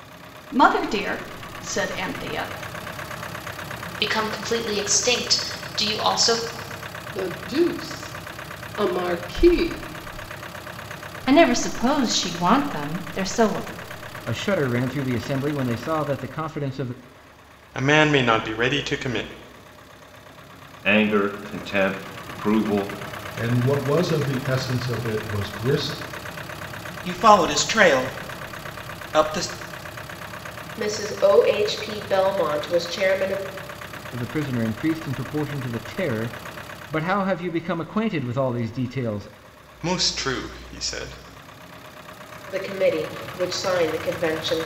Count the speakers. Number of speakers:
ten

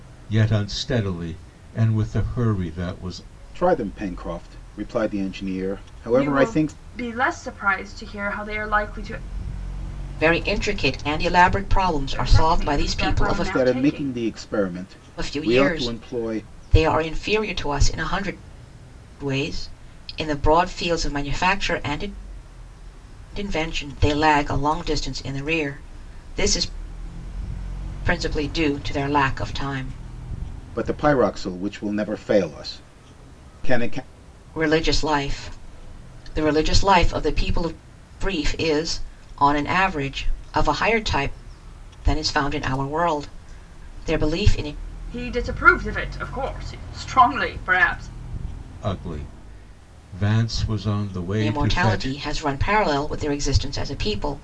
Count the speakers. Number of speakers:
four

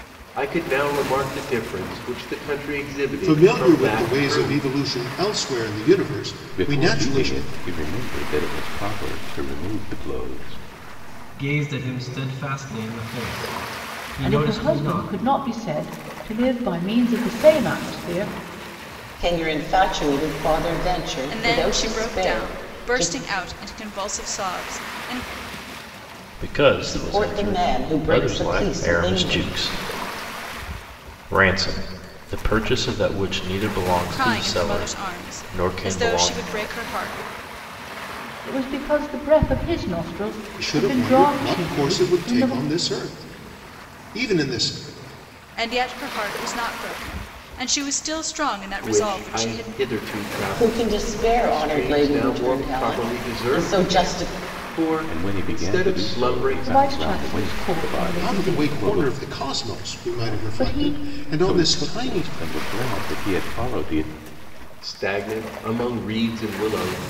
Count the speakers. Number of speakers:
eight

